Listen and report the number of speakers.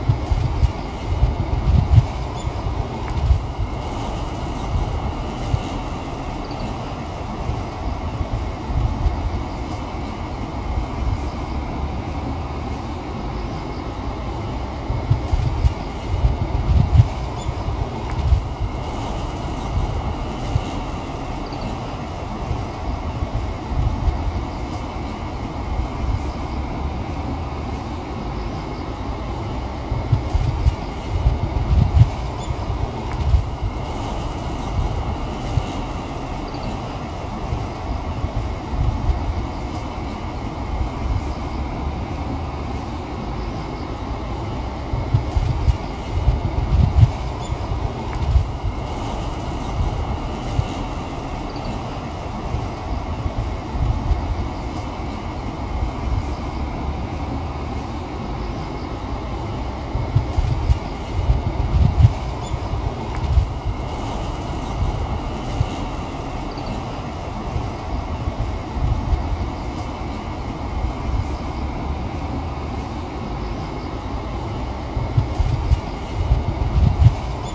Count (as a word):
zero